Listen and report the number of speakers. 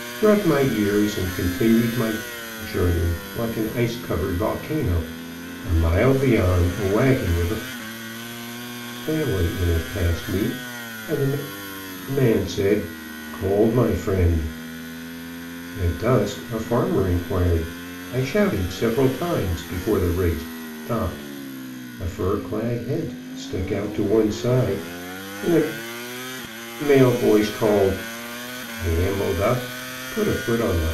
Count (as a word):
one